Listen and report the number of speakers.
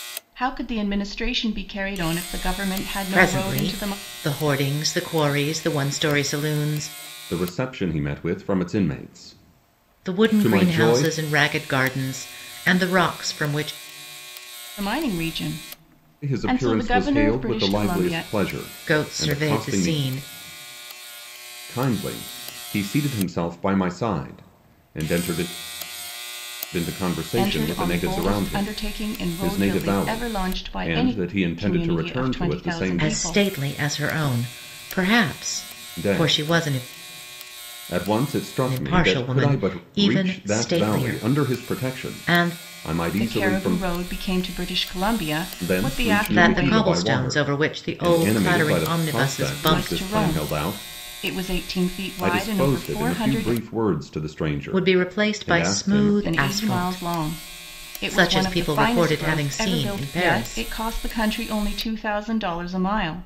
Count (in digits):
3